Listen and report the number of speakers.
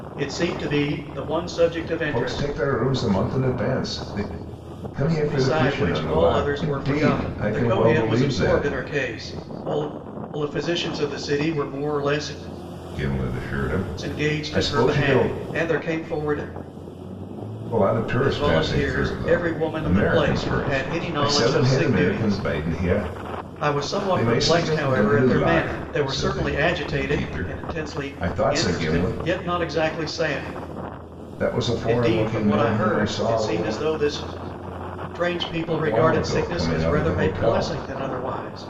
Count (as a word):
two